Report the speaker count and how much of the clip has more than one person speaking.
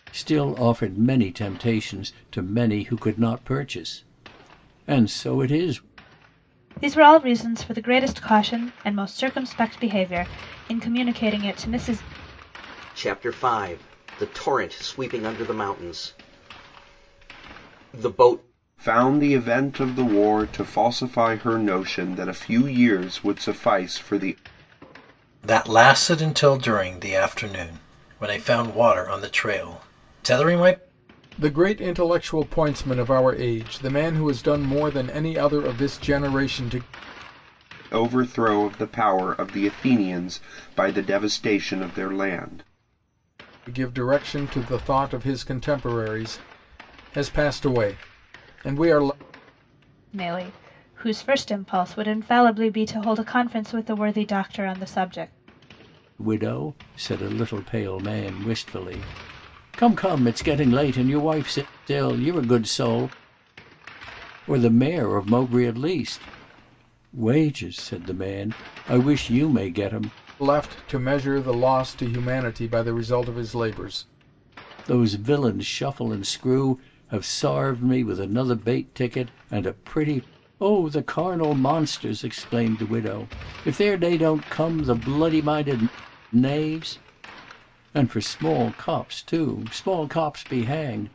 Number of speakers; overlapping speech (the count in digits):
6, no overlap